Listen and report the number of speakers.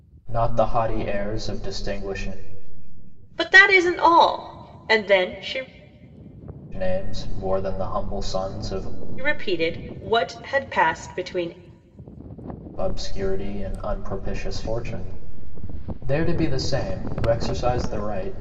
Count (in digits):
2